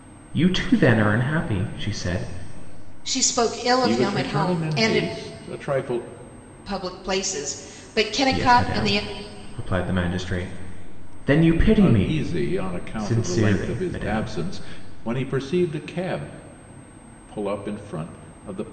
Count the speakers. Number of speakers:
three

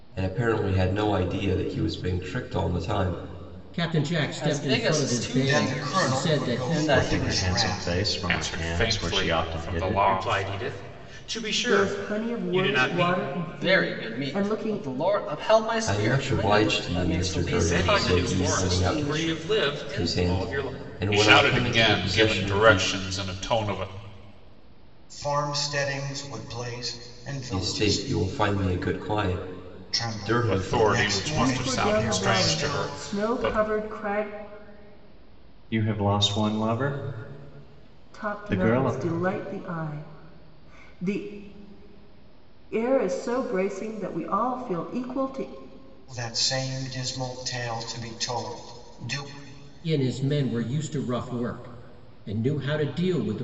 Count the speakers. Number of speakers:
eight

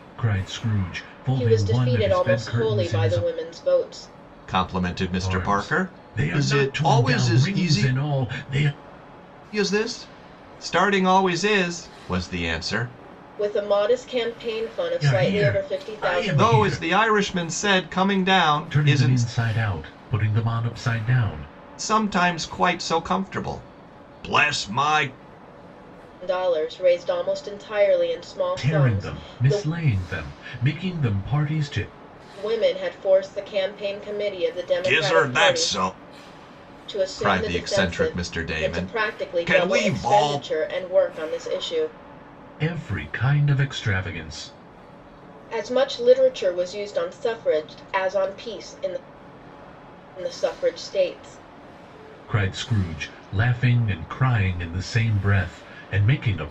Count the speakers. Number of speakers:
three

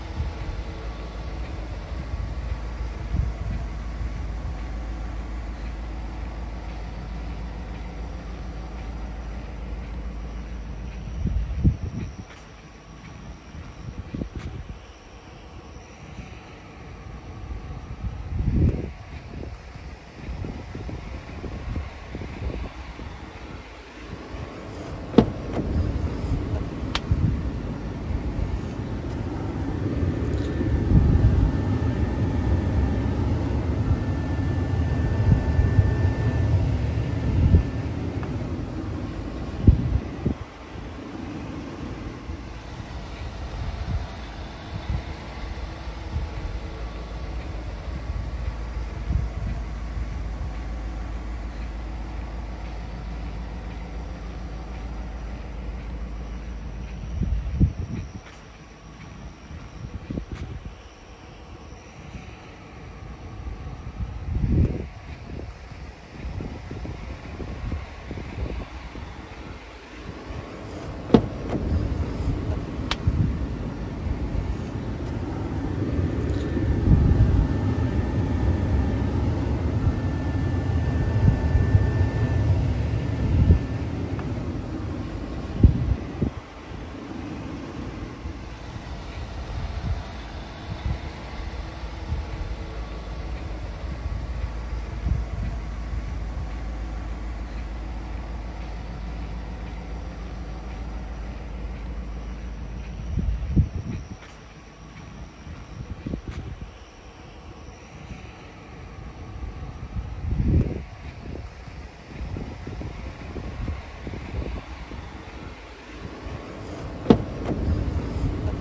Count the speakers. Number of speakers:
zero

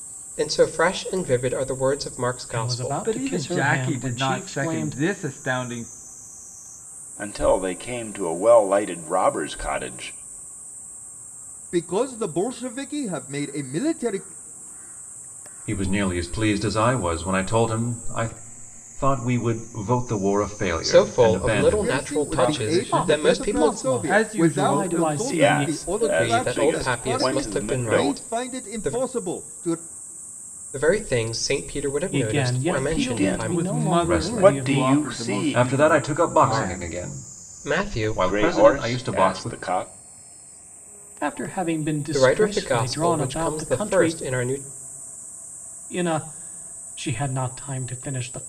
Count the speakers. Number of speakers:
six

